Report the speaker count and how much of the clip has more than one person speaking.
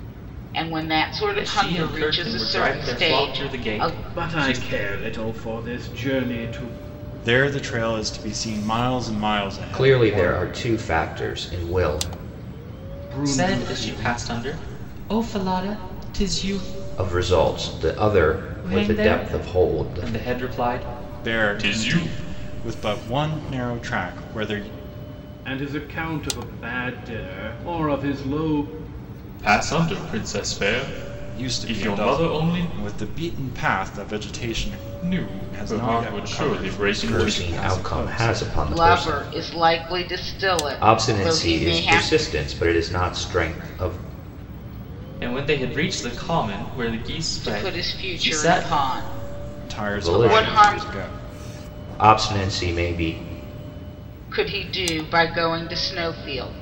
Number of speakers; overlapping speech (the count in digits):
5, about 29%